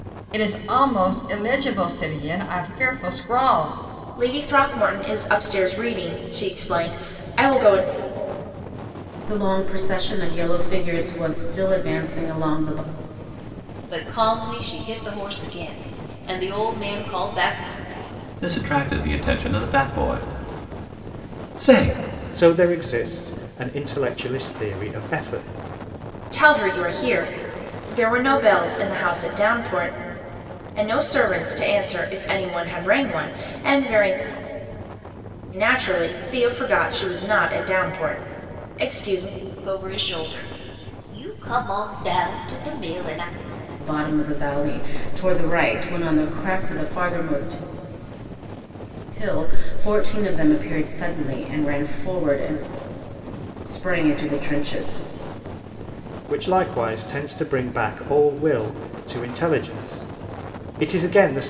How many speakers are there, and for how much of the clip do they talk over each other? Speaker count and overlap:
six, no overlap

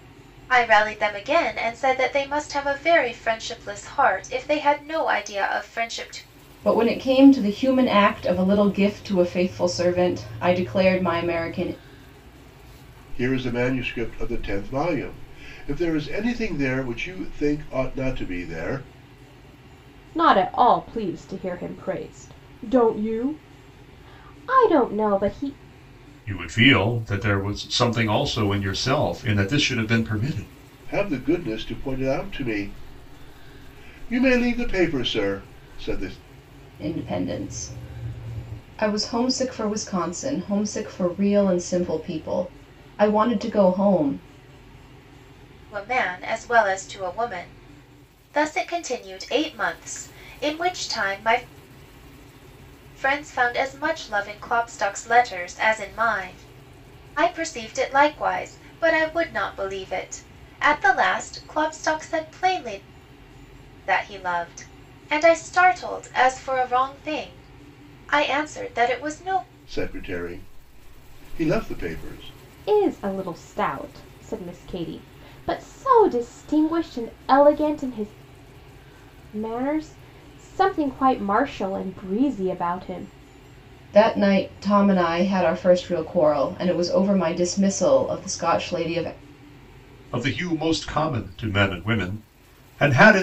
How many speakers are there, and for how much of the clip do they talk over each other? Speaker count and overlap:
five, no overlap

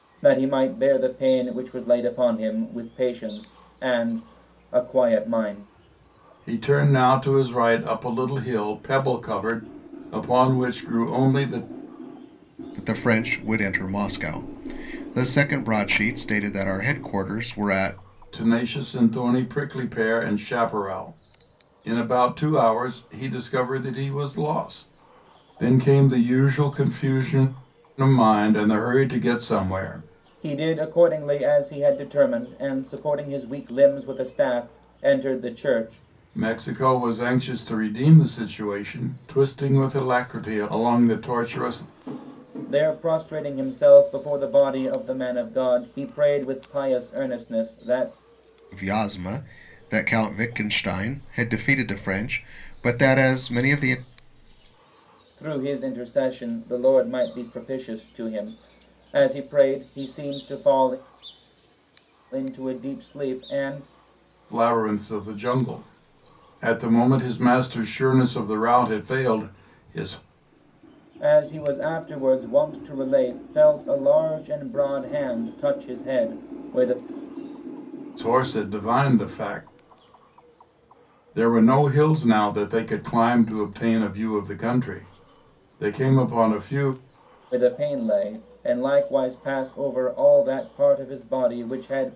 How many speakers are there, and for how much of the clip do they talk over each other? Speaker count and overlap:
three, no overlap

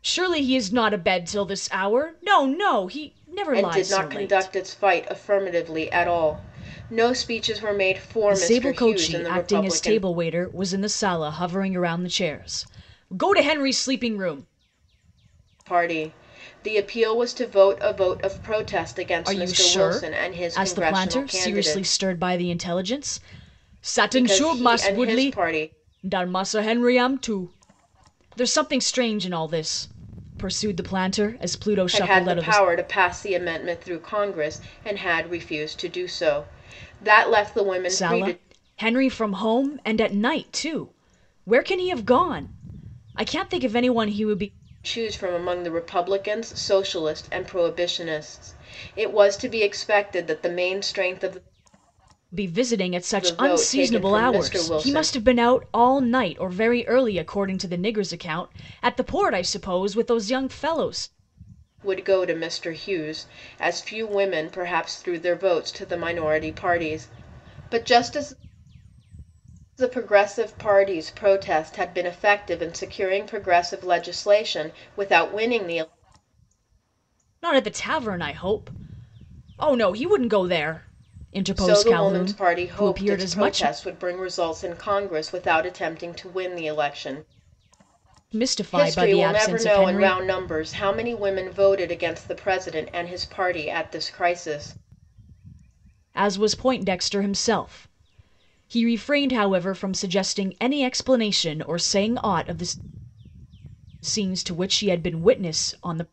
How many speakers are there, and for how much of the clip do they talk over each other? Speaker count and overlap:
two, about 13%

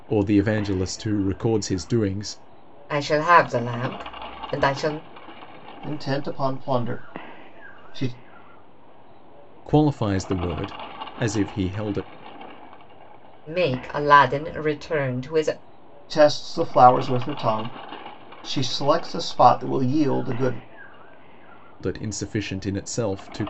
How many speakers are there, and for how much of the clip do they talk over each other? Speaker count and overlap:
three, no overlap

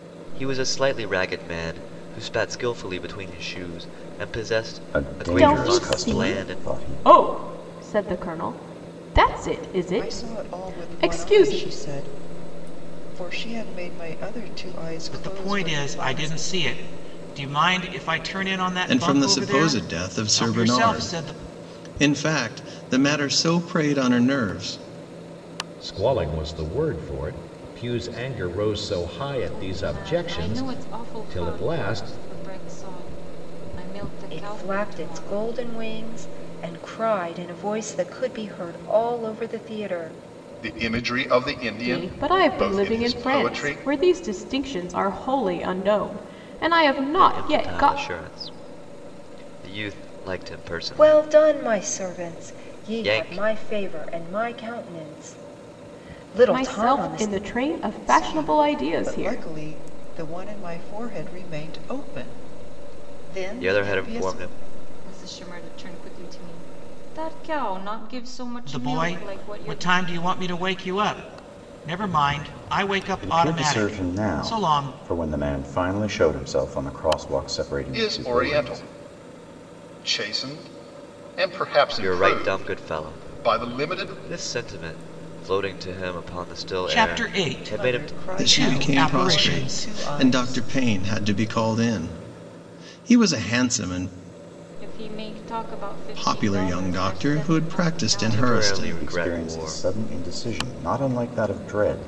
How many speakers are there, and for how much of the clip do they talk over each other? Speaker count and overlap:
ten, about 34%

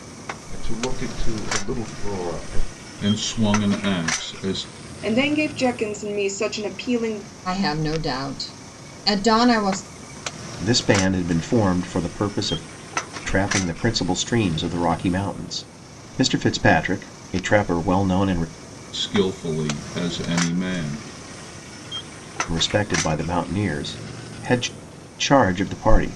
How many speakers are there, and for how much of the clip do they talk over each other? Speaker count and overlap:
five, no overlap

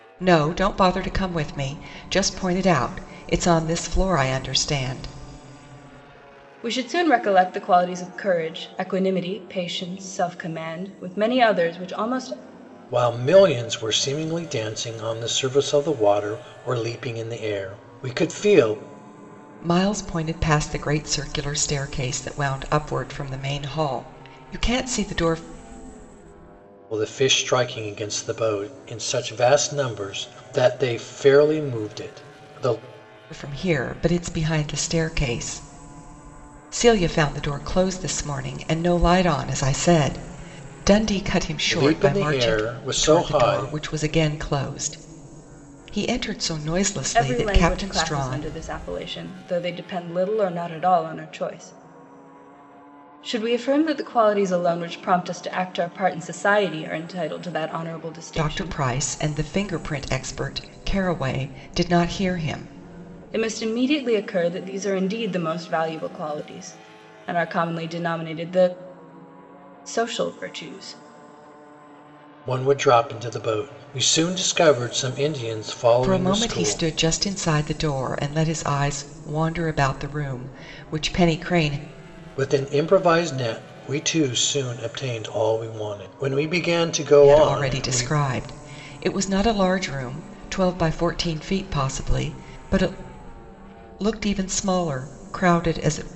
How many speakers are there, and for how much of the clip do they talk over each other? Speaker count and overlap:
three, about 6%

